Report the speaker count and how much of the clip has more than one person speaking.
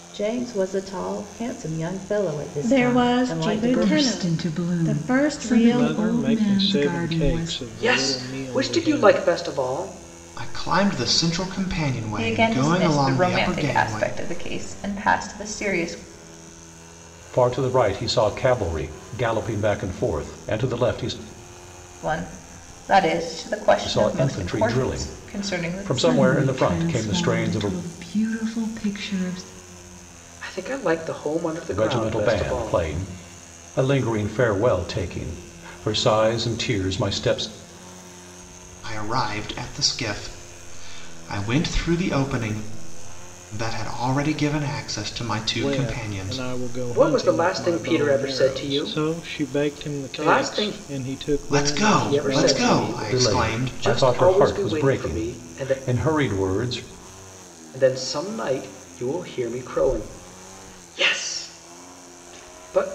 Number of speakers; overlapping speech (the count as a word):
eight, about 36%